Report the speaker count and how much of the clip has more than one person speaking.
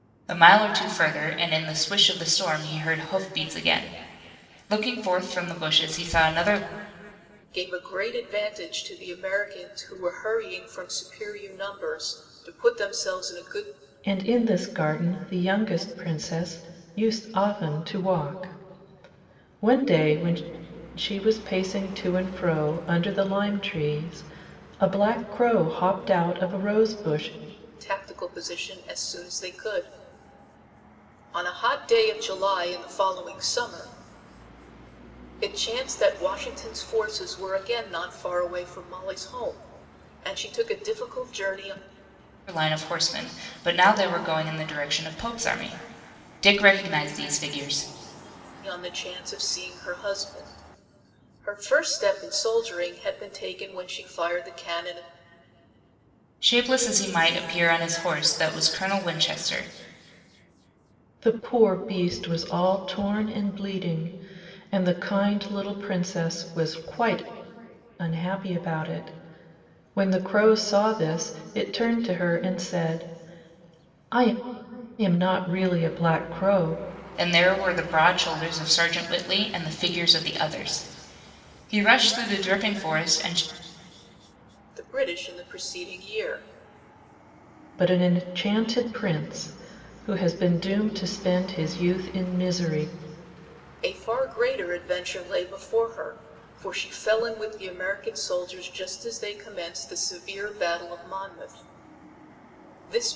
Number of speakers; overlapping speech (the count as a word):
three, no overlap